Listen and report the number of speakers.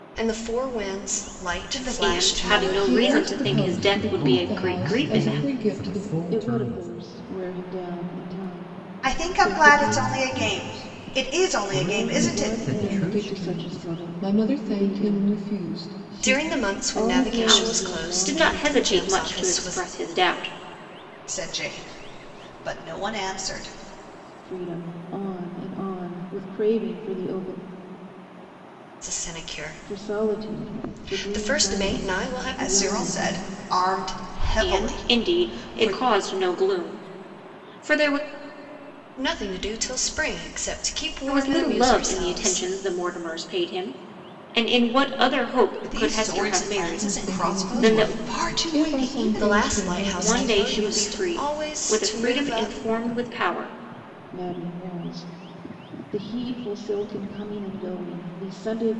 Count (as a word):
six